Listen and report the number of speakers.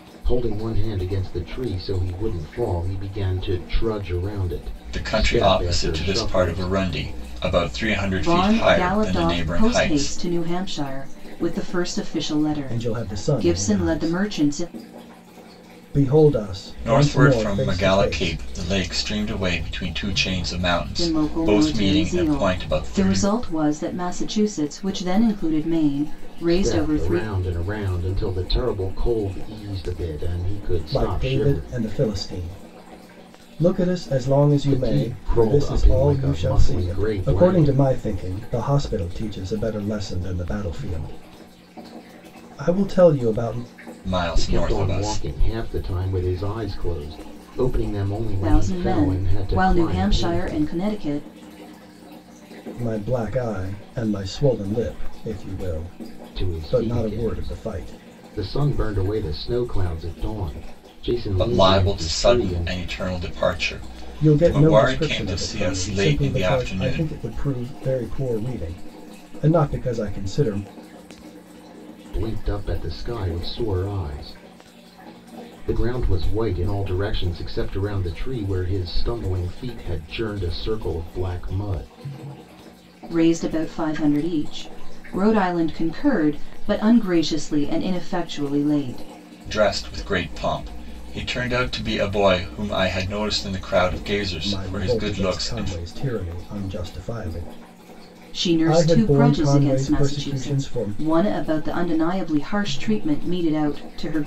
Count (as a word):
four